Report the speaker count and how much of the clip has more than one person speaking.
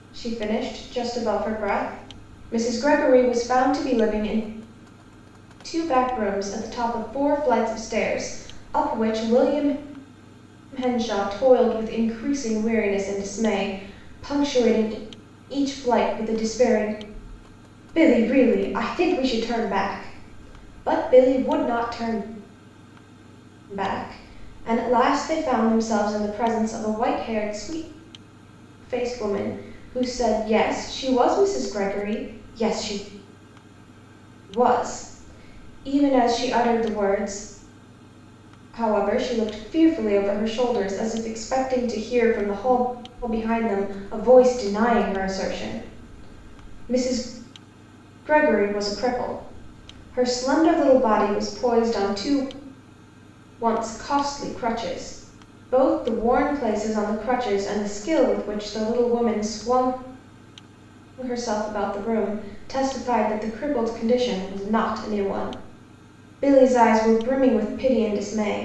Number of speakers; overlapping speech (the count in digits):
1, no overlap